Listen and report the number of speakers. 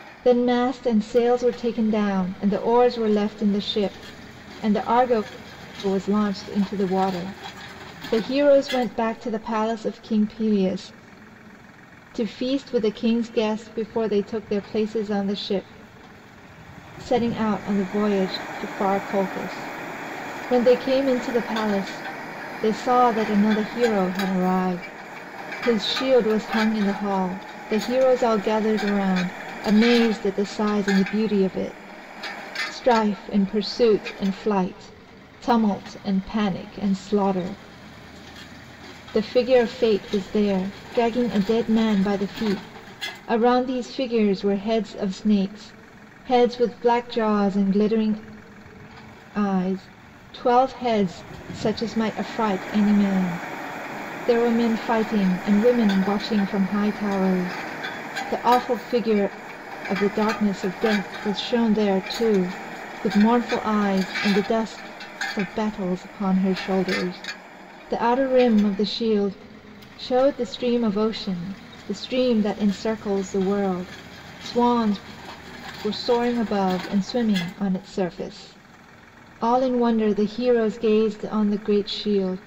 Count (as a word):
one